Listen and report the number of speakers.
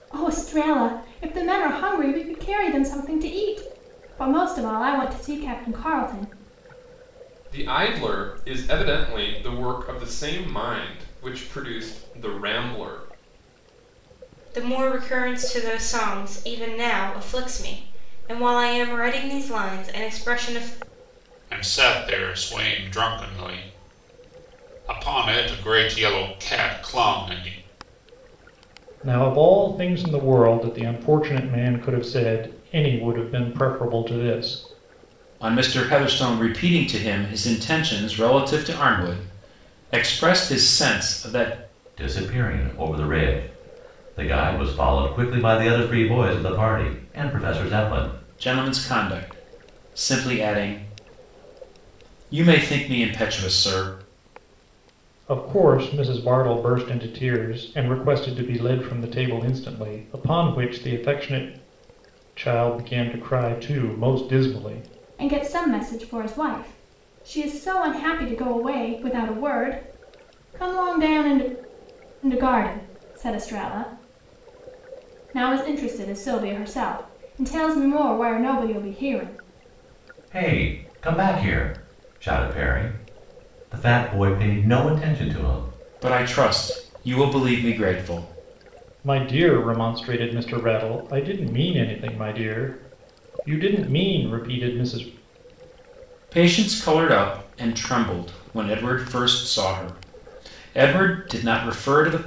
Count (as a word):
seven